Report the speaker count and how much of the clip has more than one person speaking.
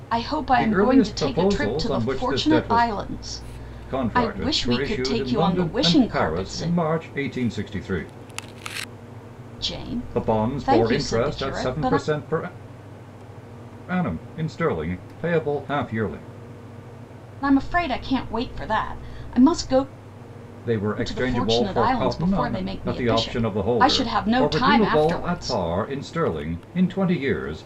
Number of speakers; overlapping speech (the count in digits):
2, about 41%